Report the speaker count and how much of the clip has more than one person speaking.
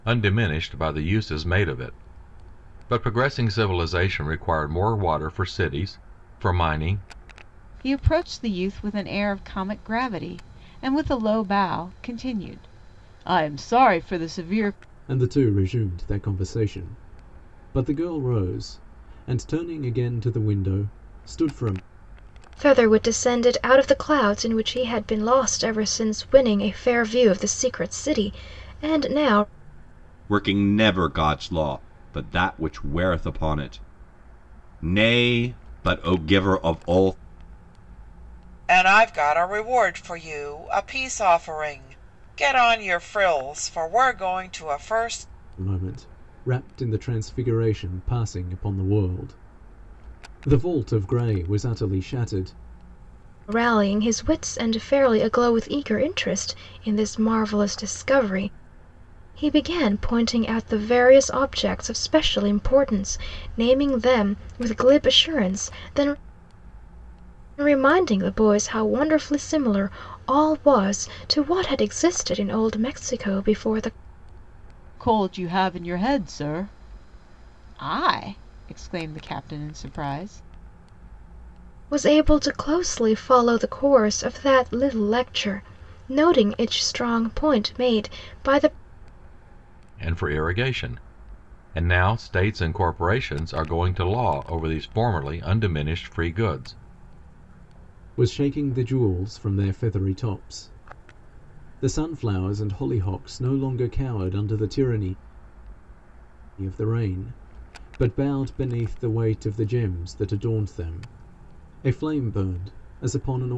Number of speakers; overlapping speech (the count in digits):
6, no overlap